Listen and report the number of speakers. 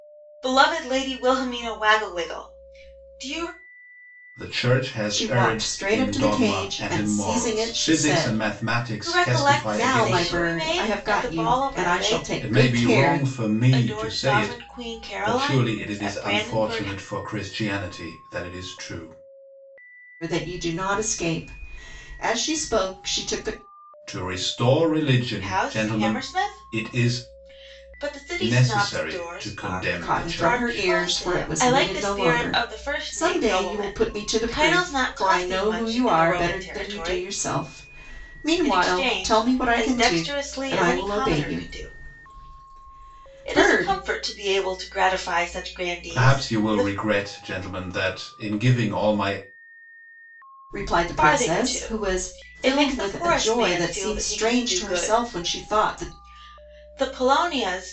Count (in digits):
3